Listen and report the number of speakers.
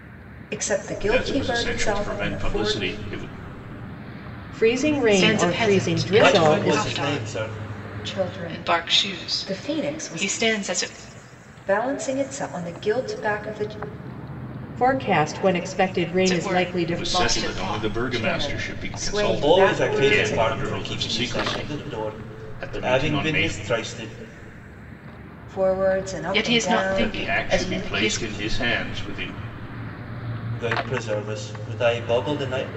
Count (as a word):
five